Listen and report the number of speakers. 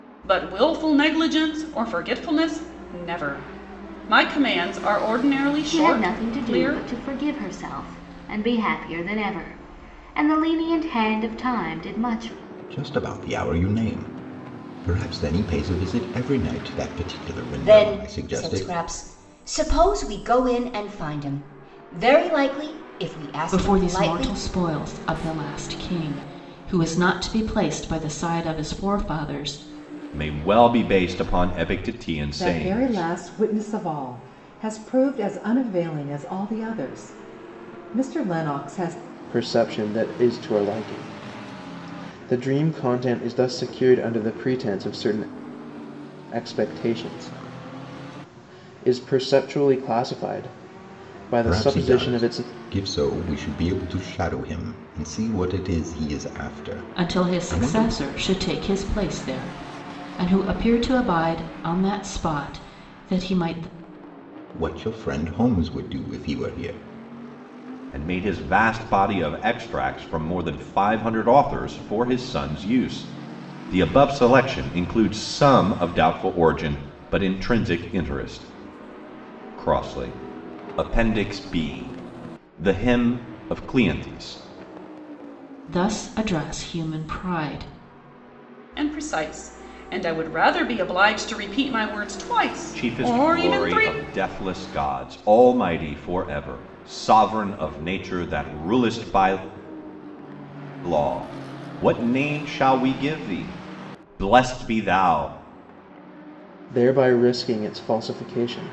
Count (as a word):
eight